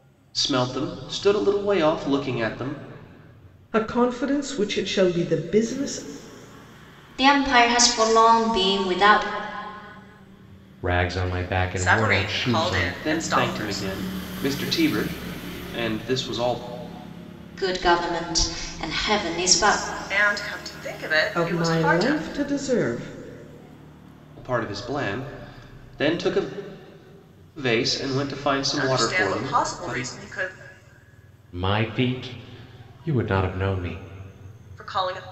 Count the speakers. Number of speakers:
5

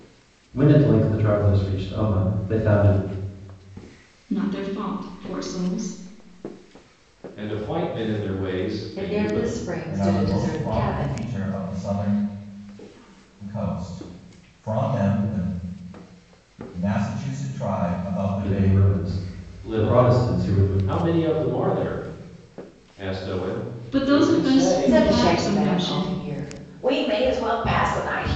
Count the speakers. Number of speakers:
5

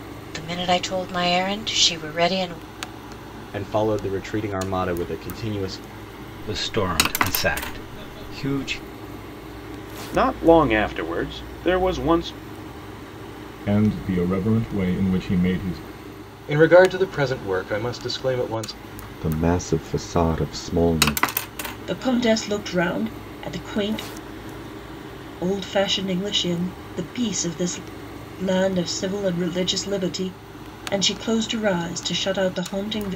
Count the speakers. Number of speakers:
8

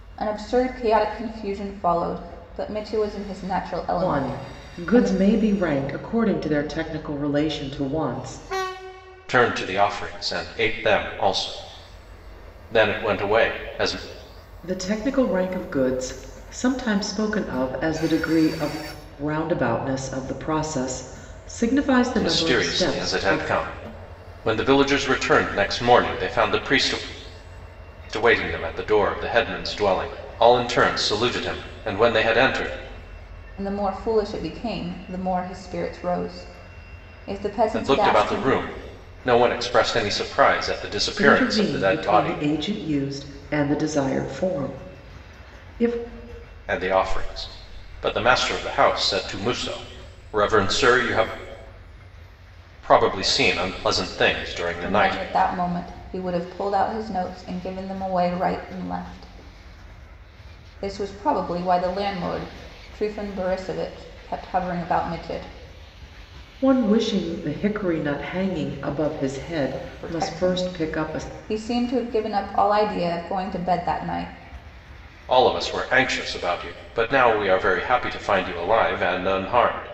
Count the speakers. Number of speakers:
3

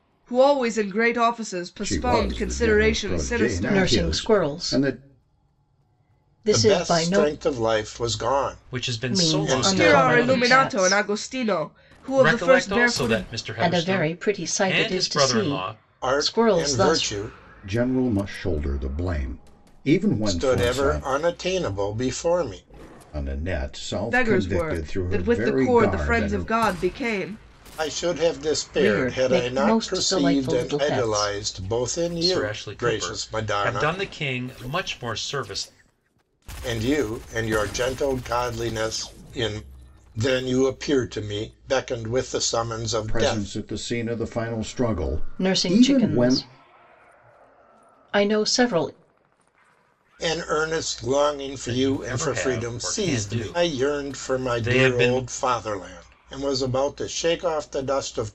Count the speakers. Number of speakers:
5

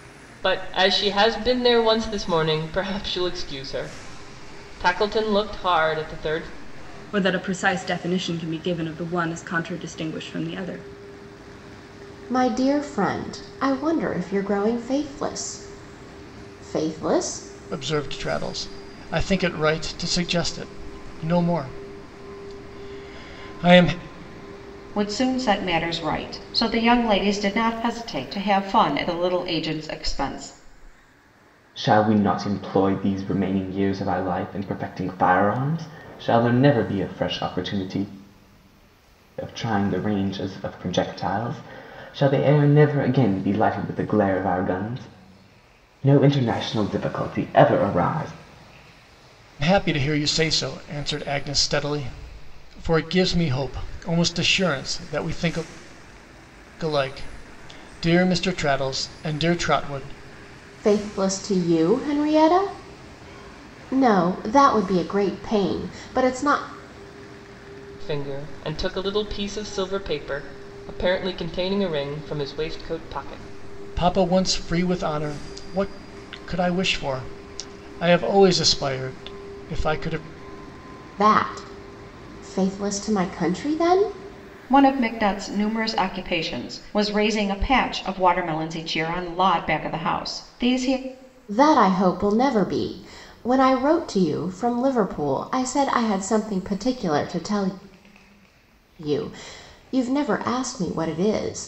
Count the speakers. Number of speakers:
6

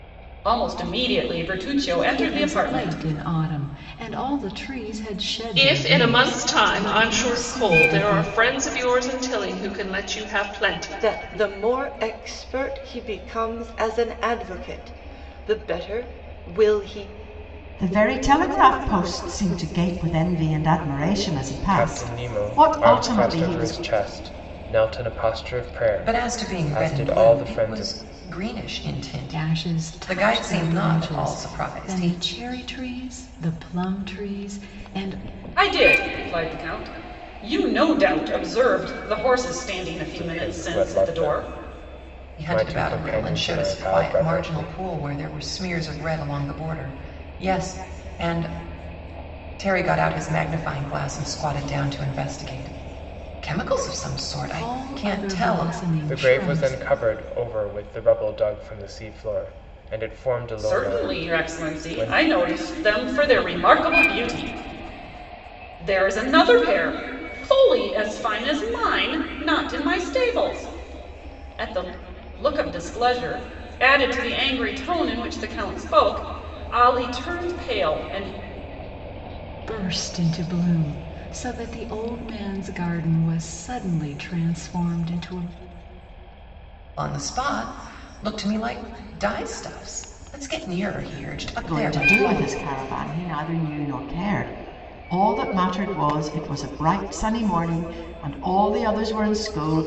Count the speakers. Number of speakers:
7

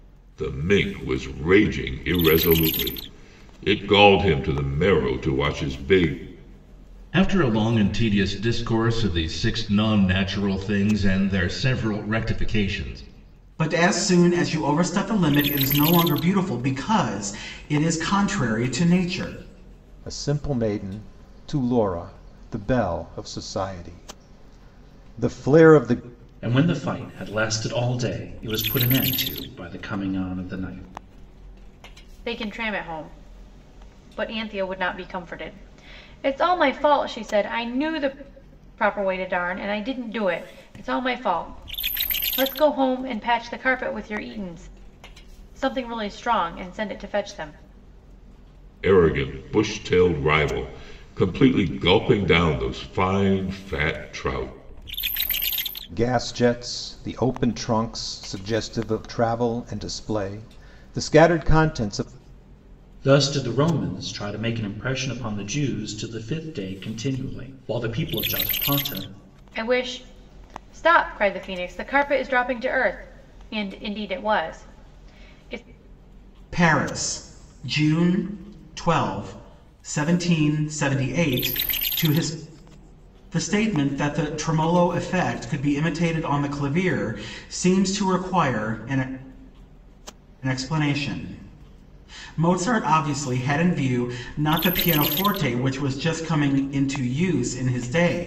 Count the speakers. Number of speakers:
6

